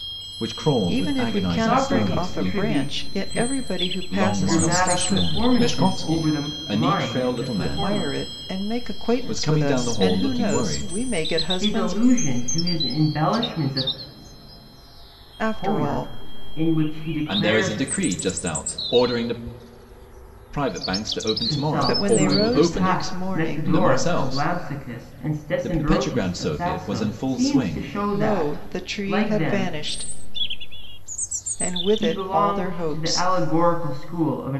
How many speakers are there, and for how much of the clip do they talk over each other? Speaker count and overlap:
3, about 56%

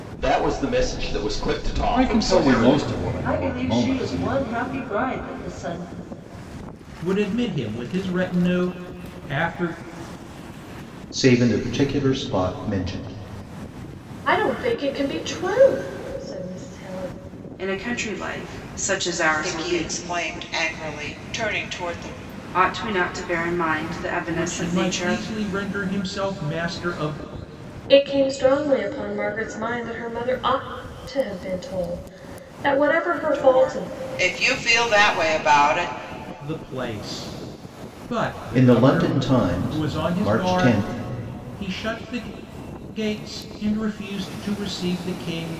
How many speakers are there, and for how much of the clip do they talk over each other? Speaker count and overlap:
8, about 13%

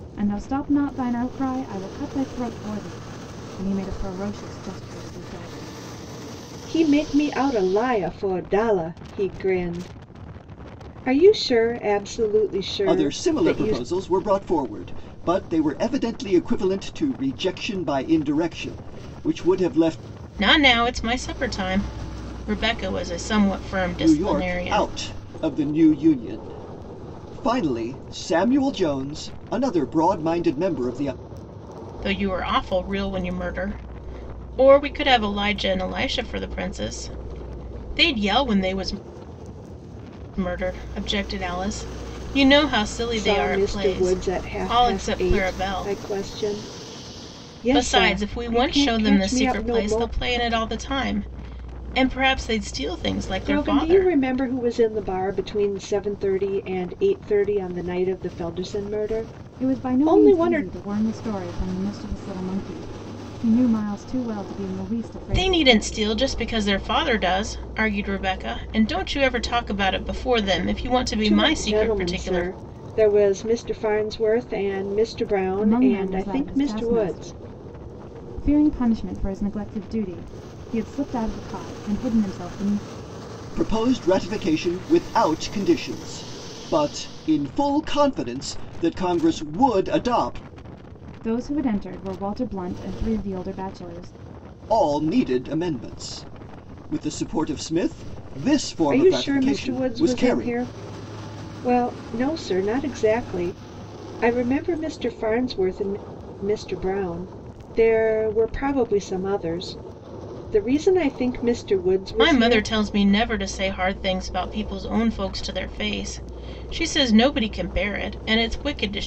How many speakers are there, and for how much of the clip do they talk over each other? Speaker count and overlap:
4, about 14%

